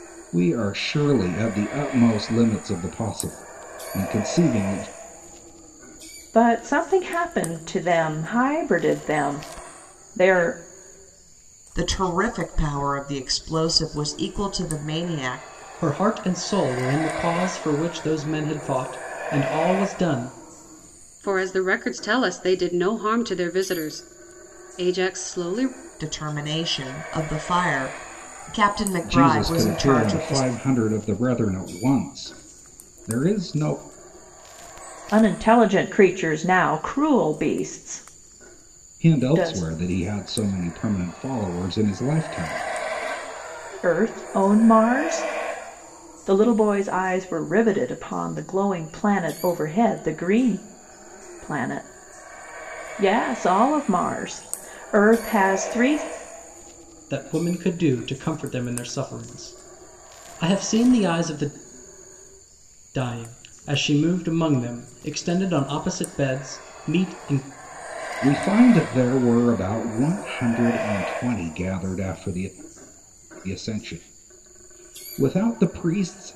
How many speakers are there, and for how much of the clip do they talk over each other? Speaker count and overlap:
five, about 3%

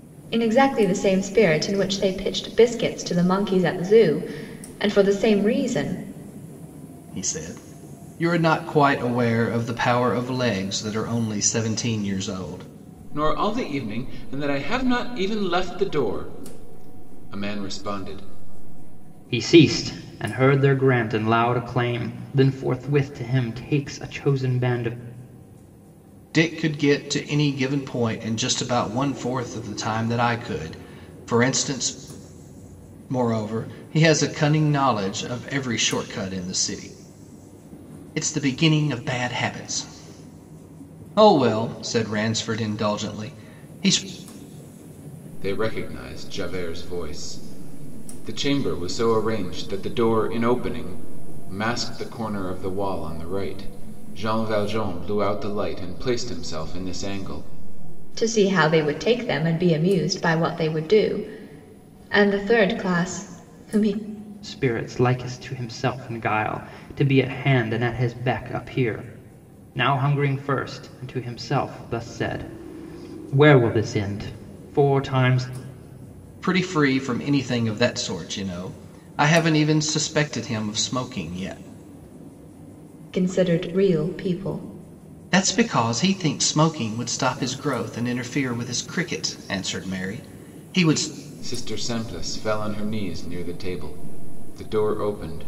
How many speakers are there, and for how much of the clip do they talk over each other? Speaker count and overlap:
four, no overlap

